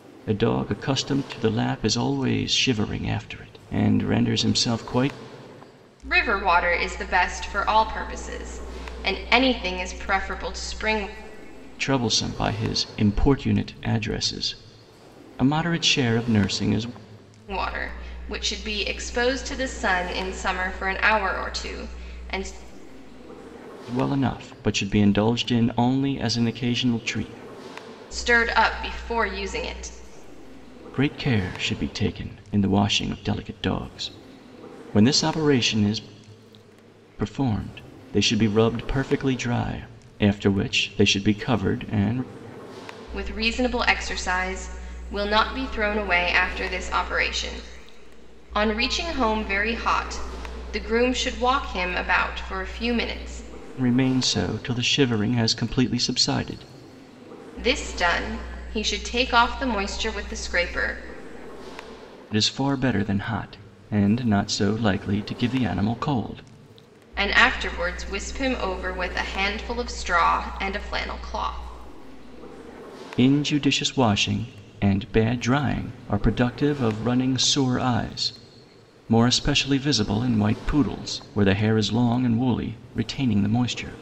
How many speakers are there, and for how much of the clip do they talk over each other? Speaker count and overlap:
2, no overlap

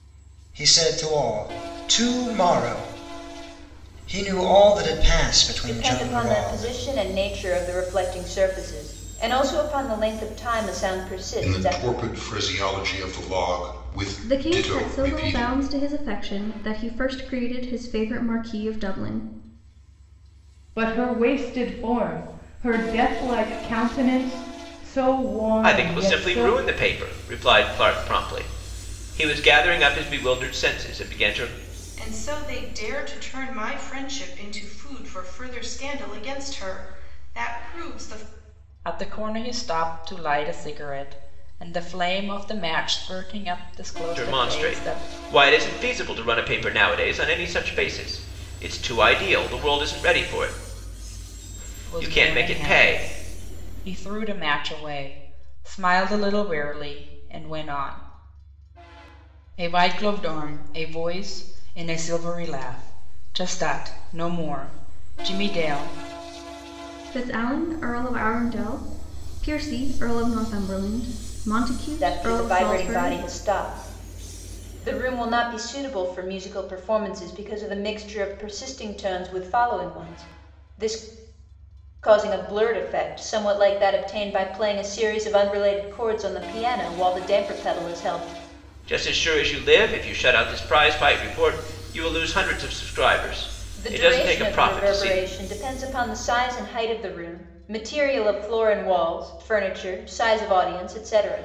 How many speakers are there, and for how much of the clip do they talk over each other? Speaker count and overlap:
8, about 8%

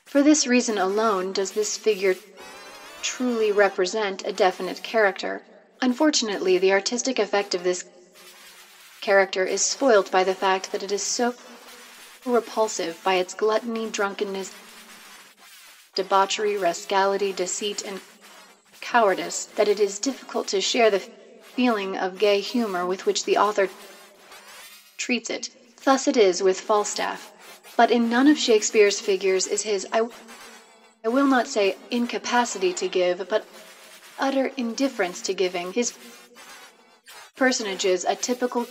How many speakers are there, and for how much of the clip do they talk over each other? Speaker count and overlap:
1, no overlap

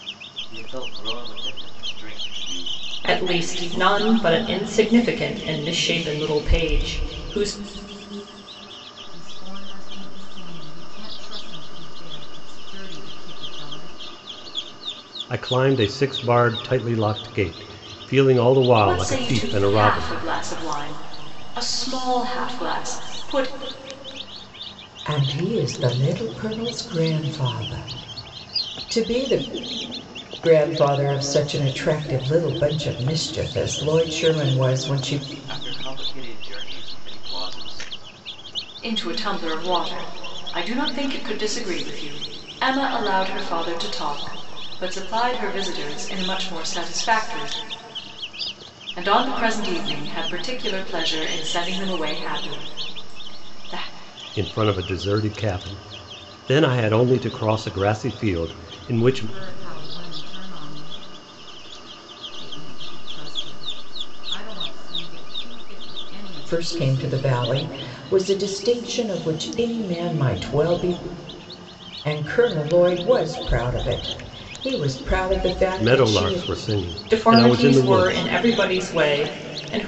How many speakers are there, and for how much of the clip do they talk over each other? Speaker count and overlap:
6, about 7%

